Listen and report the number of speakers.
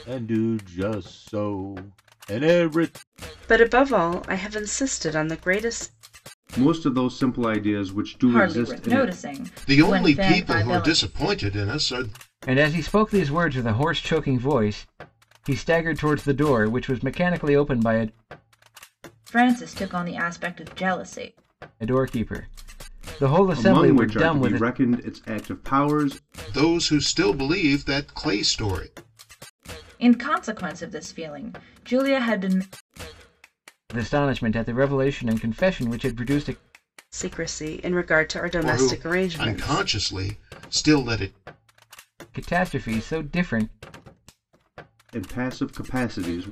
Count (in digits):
6